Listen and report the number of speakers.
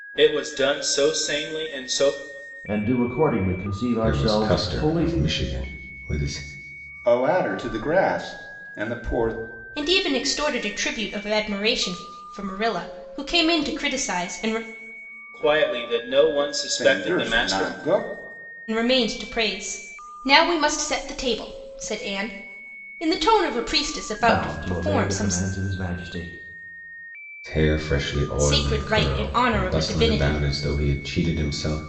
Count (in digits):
5